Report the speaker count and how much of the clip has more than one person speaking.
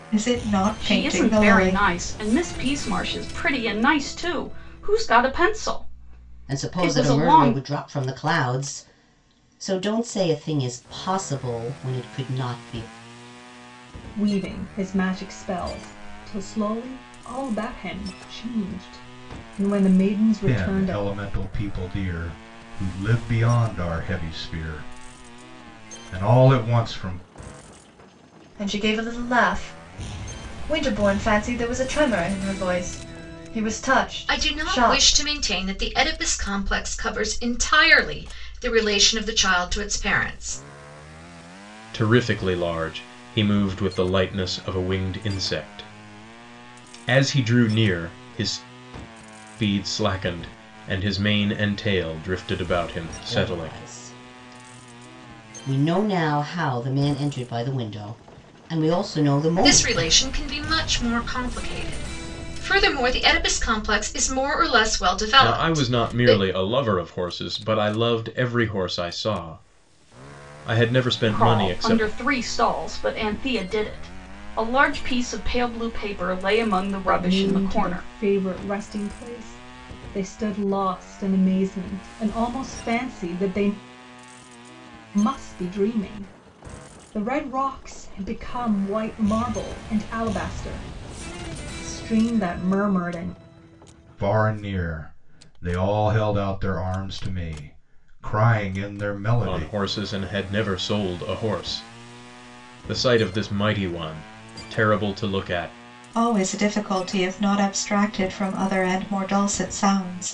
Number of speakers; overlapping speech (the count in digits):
8, about 8%